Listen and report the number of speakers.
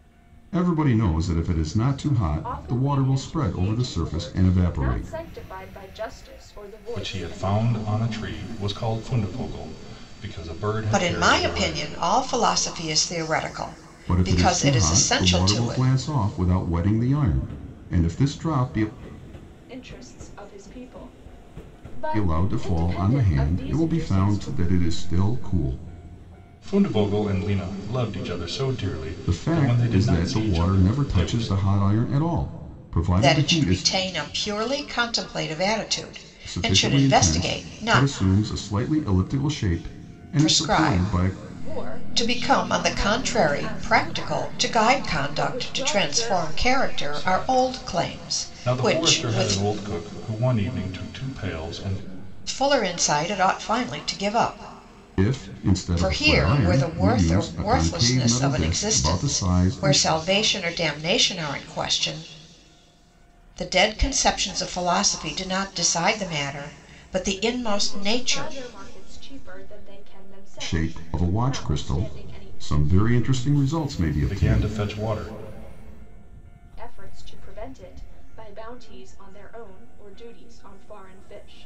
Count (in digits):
4